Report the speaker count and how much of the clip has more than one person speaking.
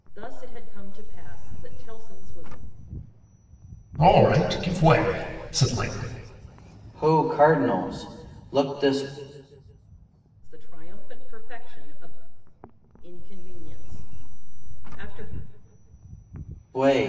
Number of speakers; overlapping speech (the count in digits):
3, no overlap